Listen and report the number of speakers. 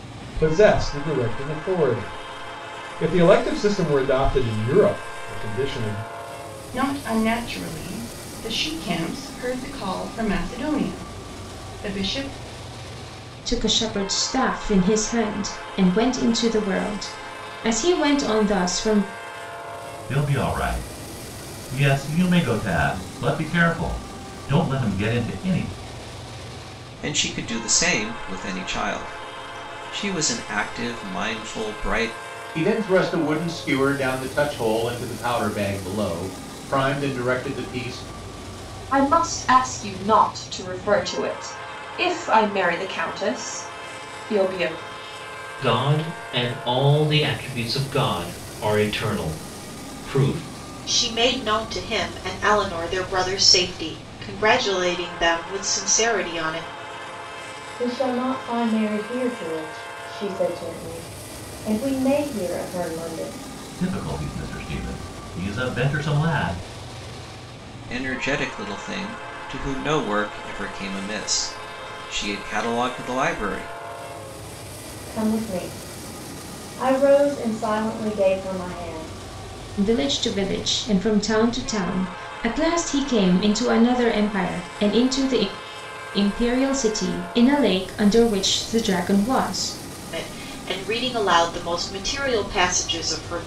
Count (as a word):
ten